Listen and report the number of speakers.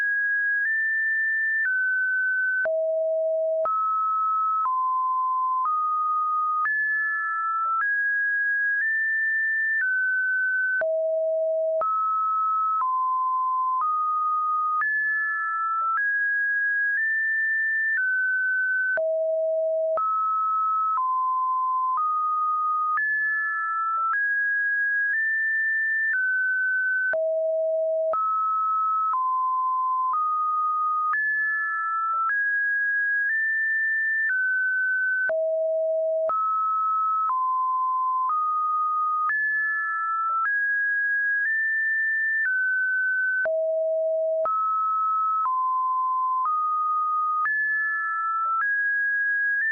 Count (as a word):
zero